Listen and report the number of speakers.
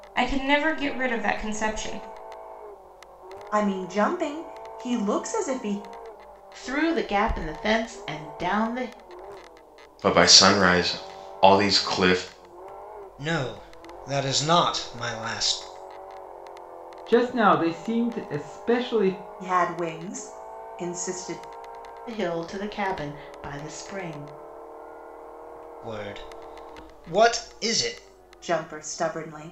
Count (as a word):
six